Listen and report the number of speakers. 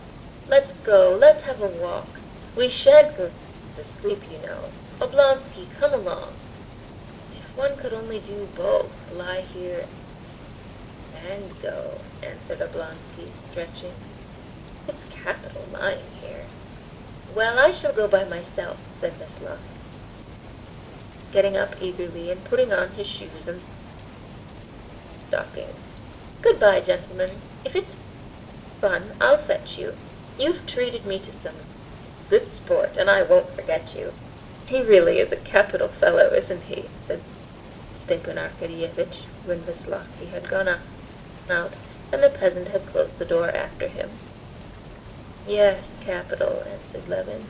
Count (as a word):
one